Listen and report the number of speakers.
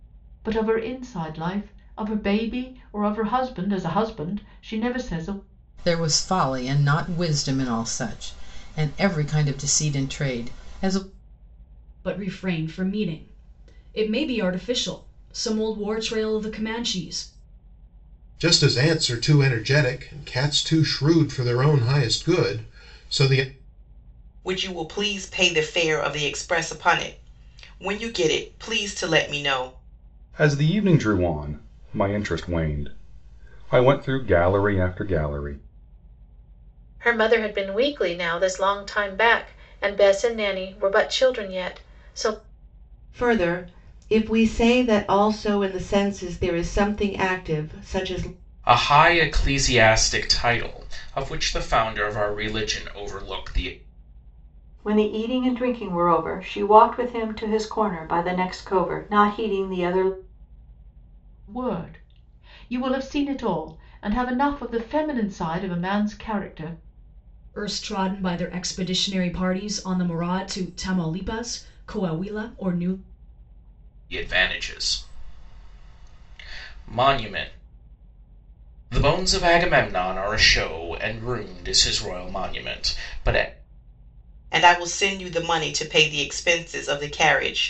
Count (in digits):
10